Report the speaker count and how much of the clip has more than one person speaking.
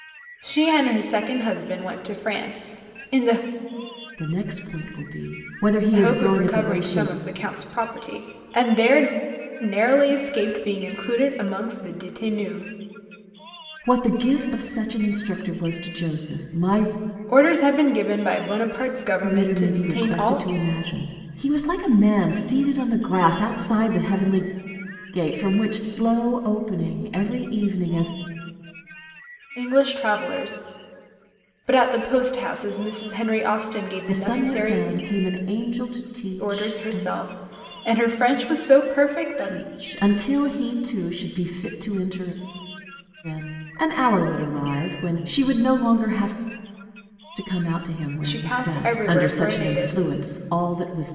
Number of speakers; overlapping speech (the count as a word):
two, about 12%